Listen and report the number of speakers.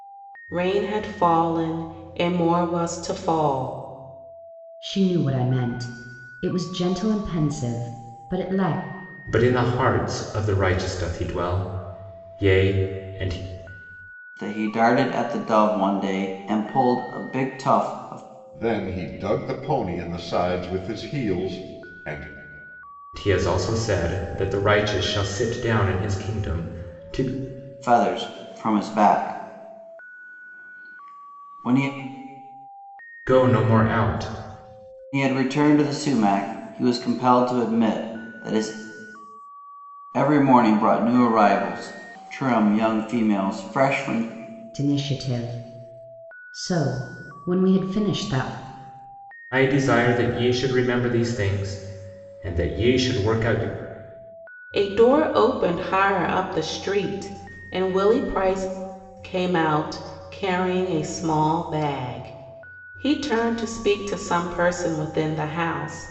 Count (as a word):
five